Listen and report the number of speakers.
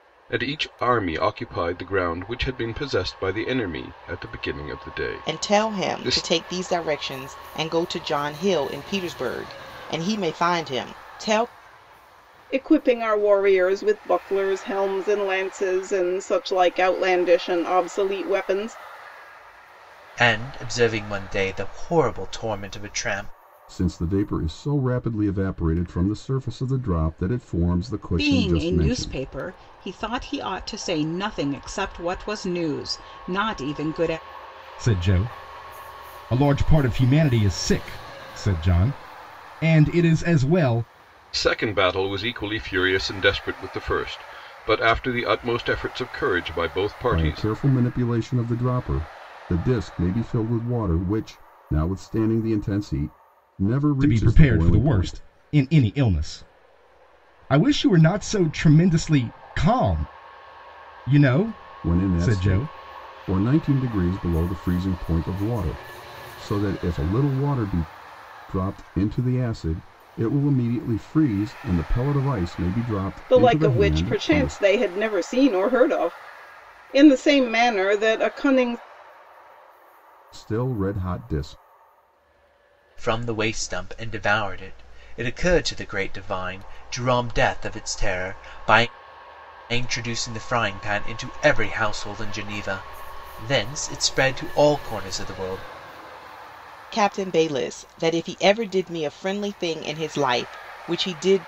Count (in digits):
7